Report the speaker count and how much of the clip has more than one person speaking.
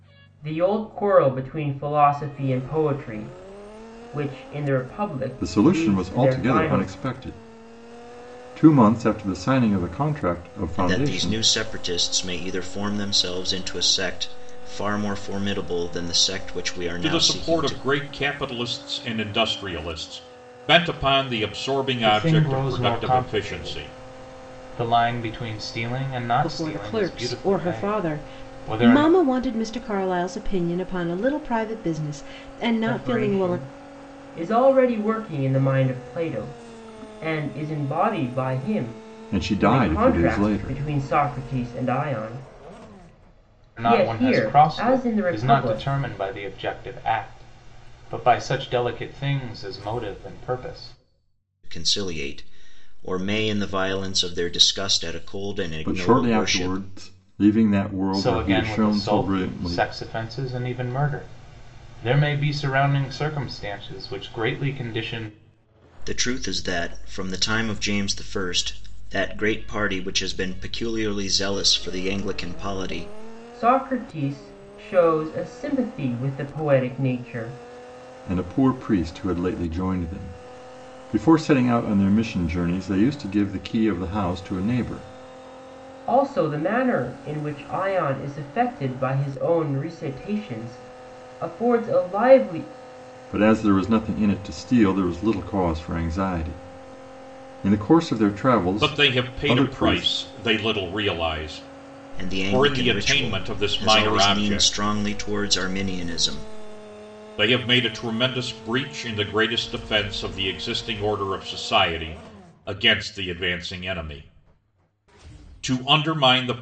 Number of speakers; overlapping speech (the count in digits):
6, about 16%